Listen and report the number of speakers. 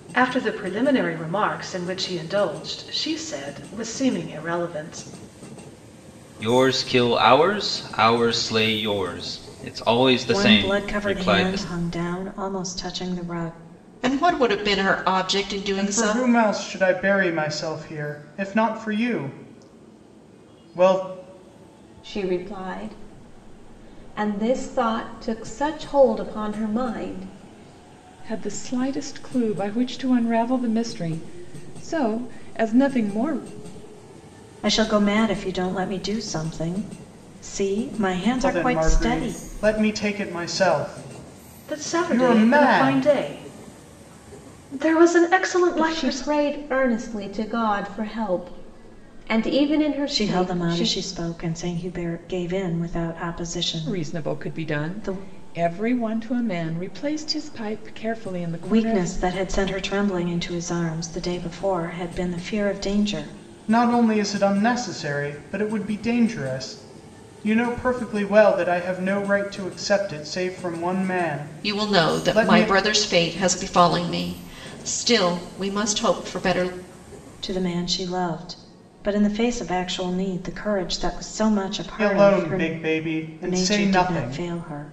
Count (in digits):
7